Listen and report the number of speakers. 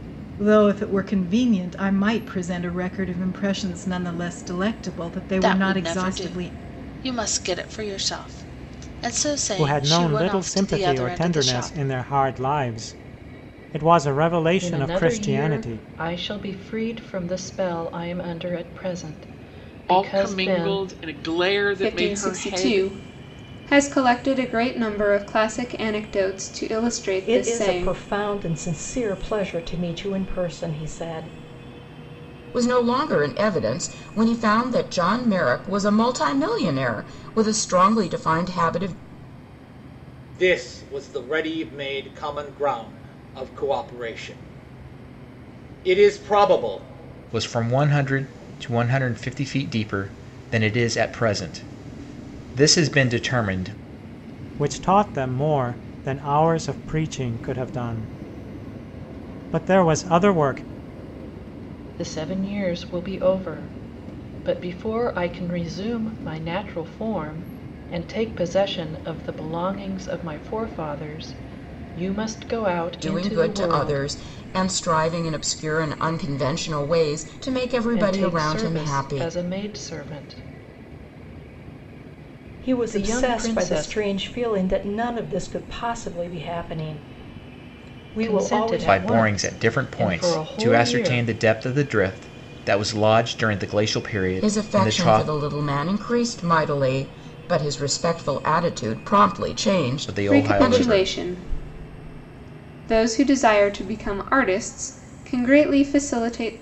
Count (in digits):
10